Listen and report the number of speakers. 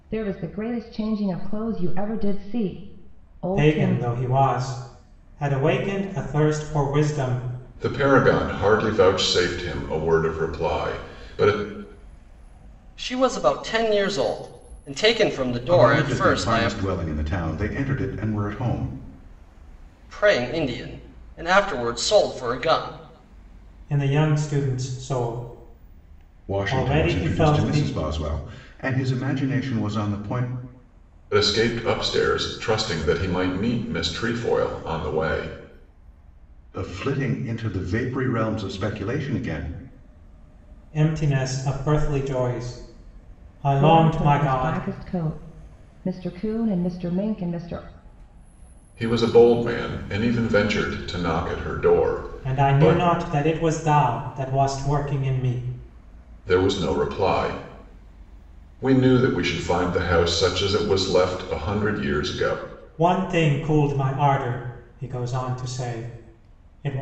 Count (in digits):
5